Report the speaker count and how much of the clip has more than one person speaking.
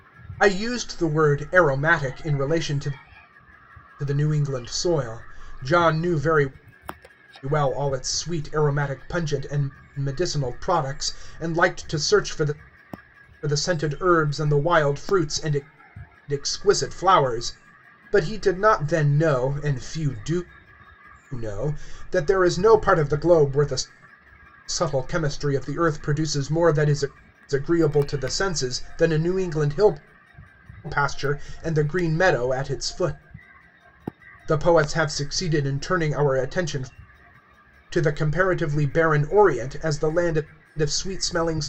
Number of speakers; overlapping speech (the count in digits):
1, no overlap